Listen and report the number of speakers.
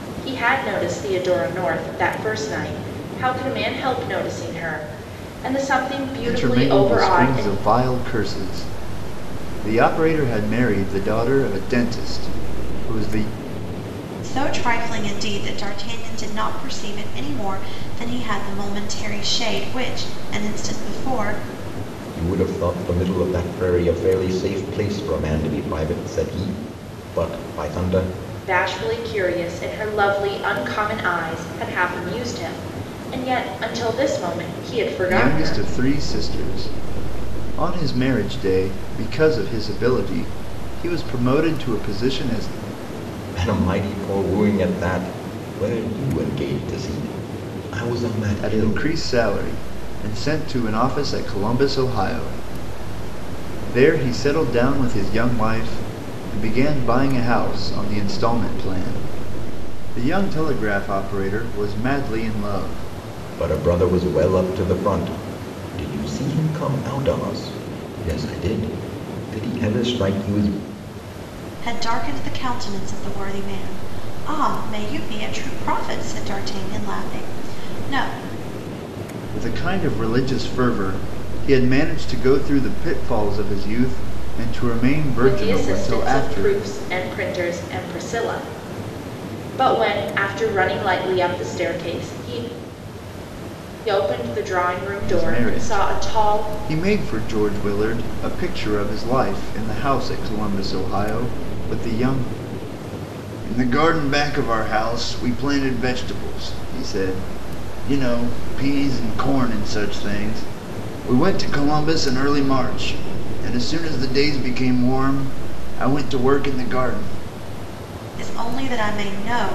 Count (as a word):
four